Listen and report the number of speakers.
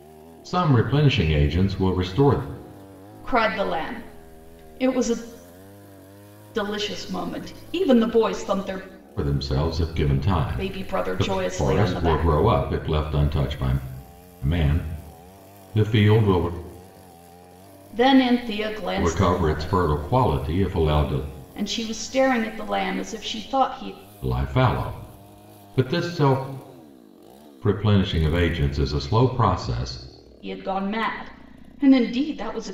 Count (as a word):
two